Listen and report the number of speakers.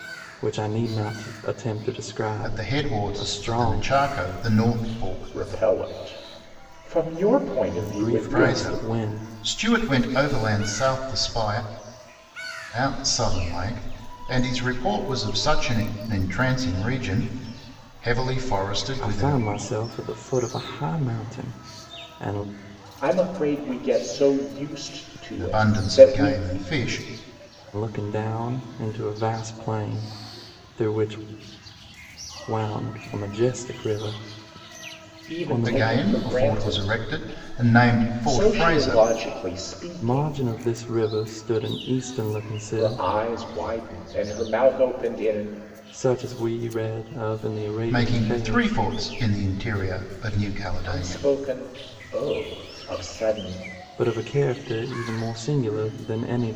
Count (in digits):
3